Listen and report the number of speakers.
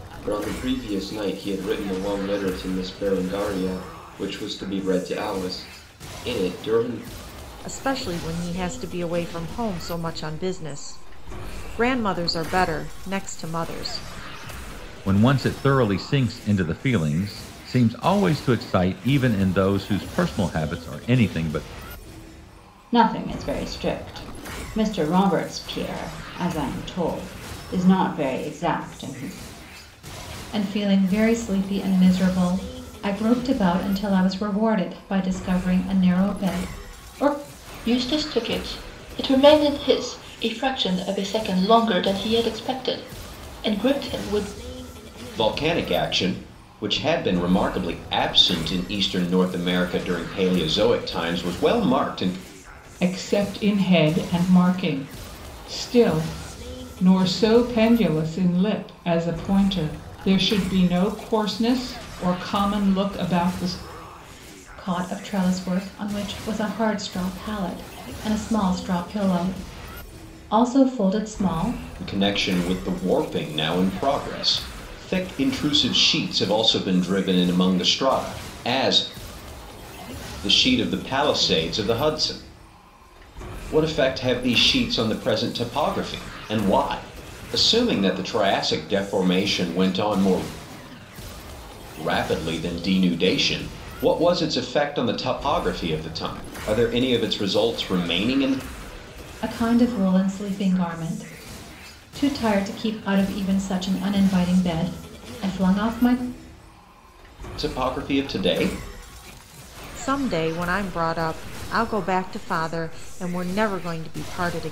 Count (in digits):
8